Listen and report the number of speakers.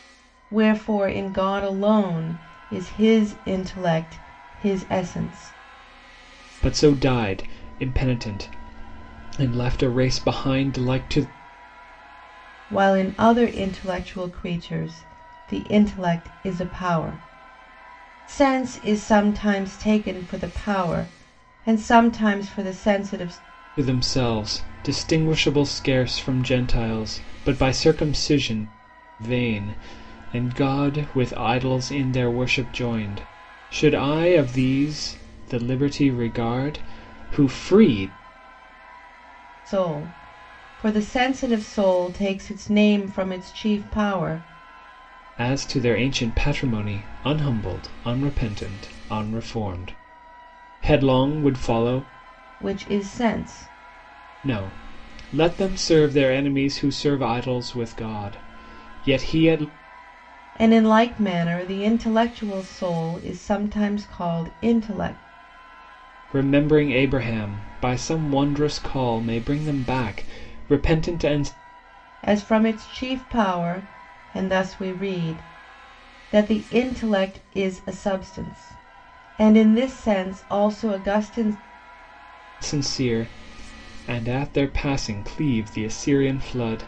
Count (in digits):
2